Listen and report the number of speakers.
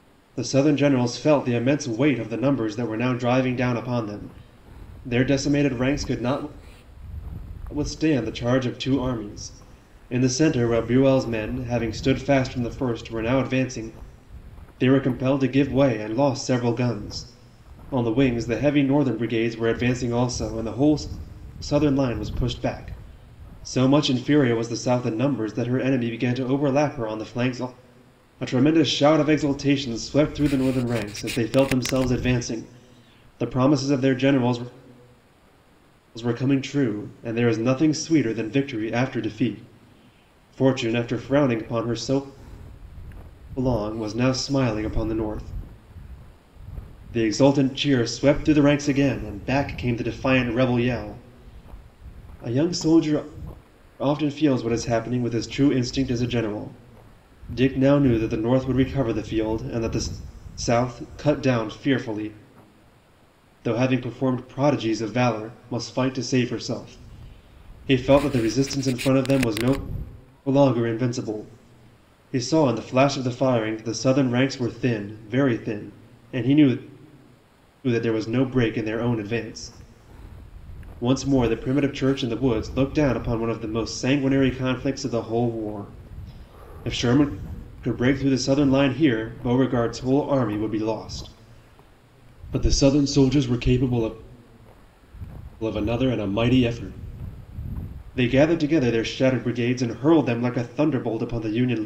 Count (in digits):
1